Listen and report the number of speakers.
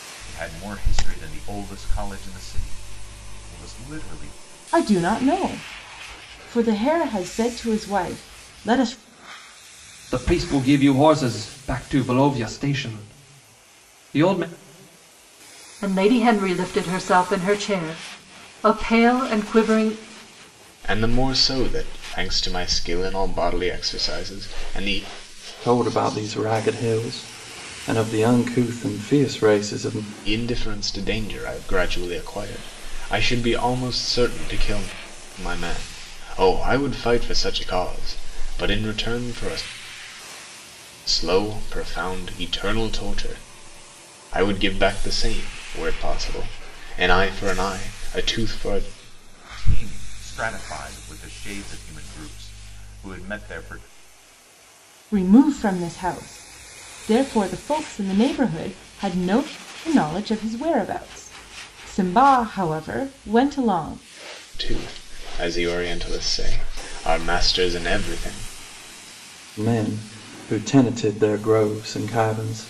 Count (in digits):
6